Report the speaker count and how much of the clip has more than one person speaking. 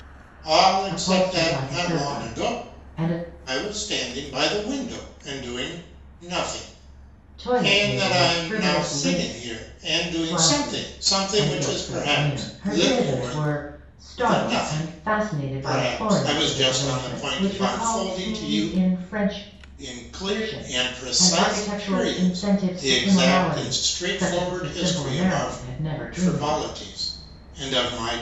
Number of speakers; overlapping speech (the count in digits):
2, about 62%